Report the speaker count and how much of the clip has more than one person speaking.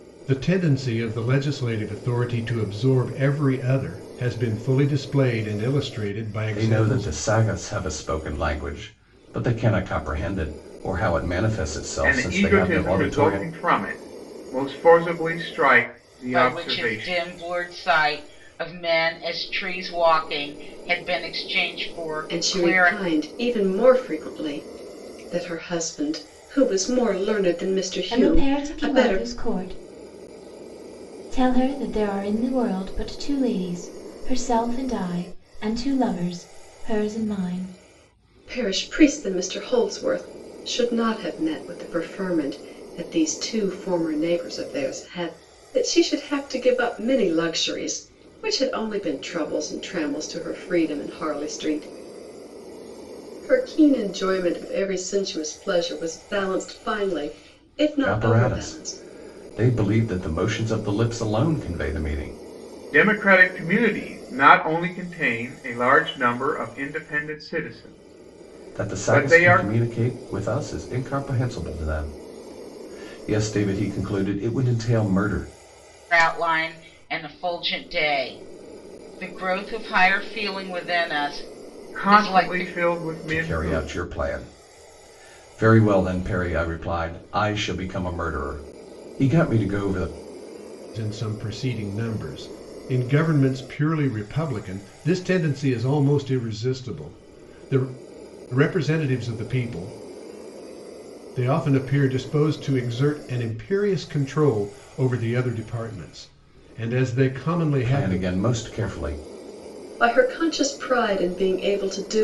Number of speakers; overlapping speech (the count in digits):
6, about 8%